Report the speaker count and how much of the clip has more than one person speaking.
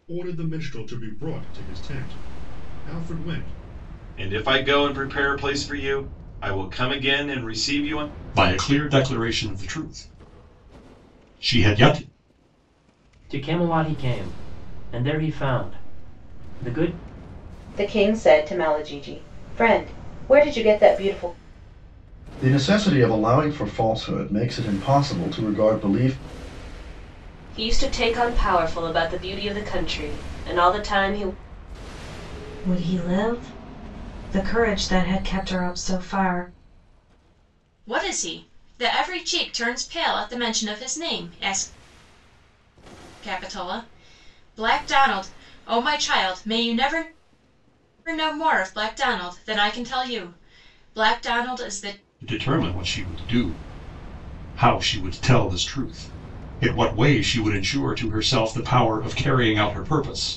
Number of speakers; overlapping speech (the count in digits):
9, no overlap